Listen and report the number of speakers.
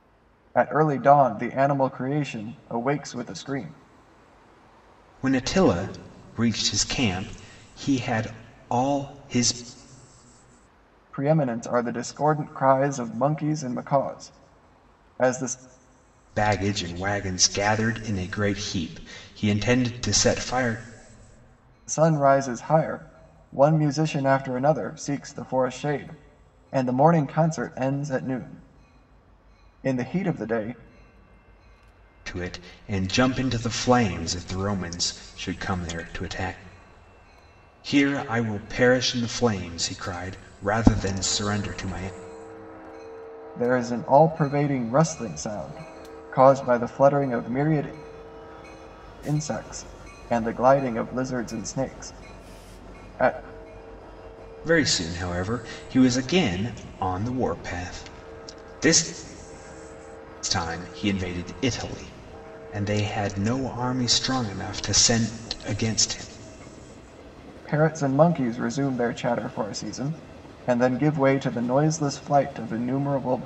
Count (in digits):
2